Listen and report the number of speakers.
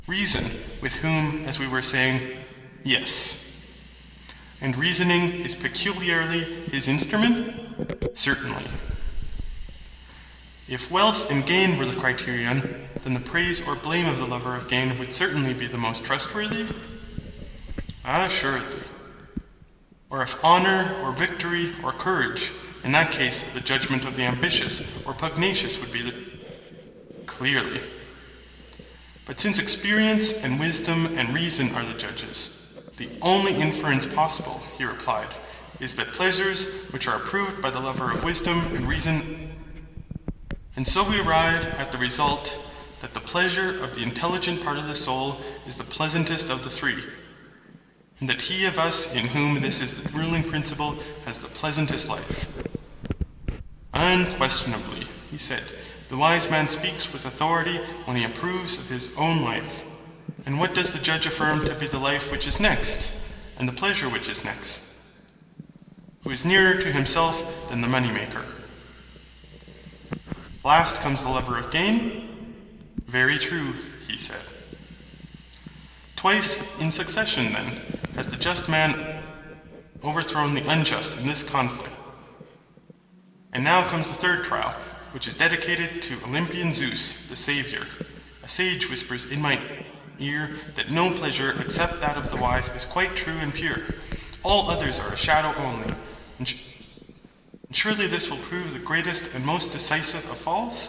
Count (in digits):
1